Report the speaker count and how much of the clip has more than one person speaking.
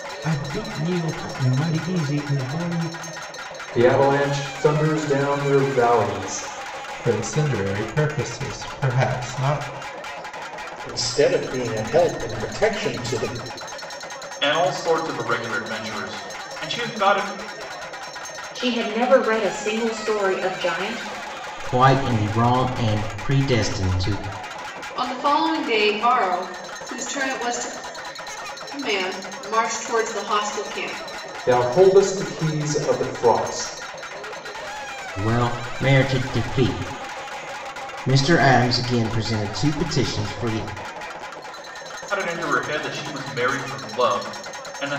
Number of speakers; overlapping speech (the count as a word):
eight, no overlap